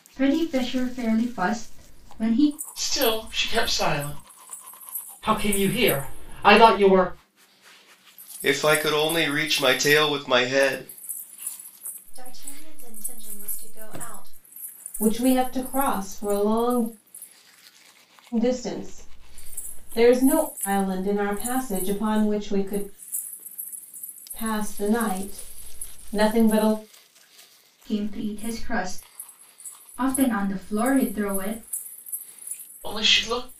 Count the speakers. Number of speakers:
six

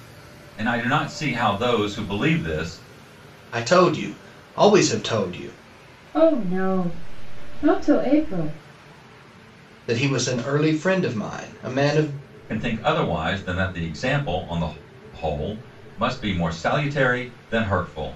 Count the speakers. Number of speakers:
three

